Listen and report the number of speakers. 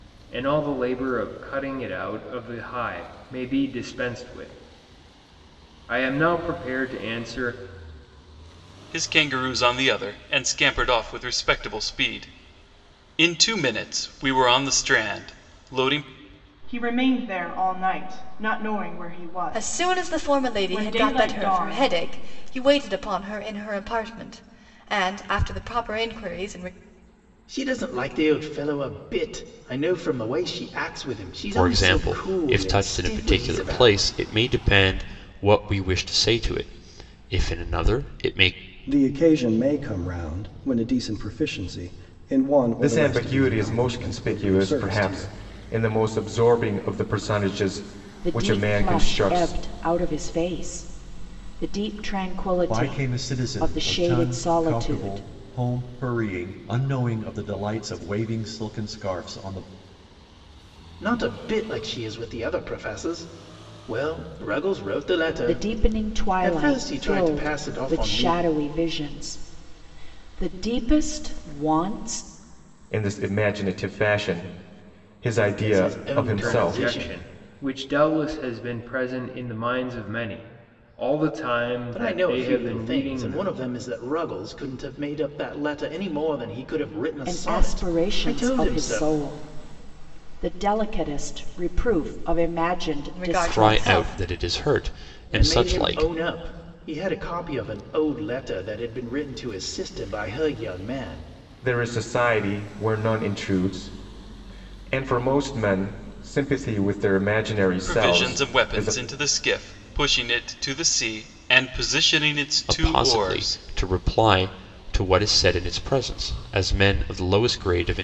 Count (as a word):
ten